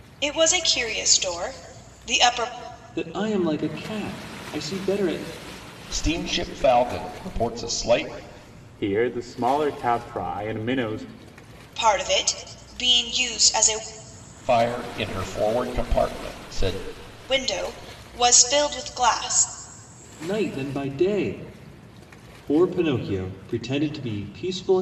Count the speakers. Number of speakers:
4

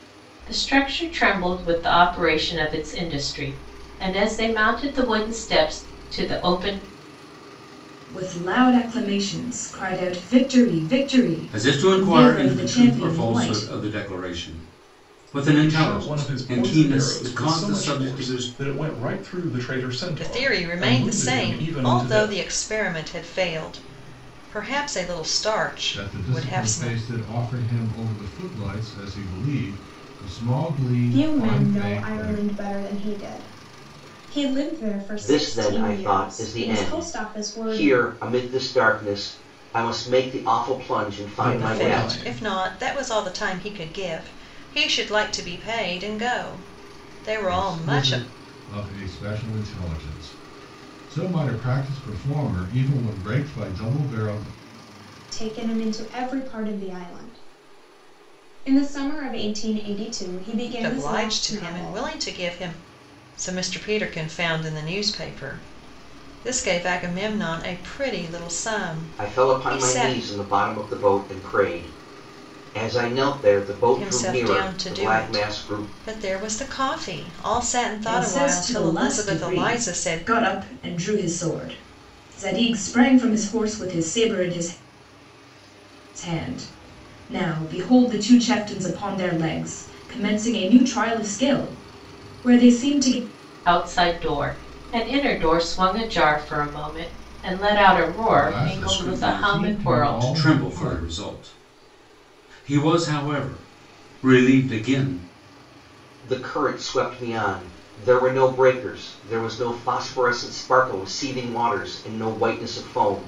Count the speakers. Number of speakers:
8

